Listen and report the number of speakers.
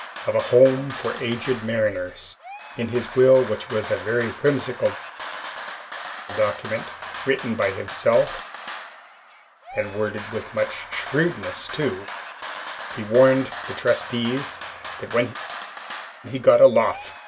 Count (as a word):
one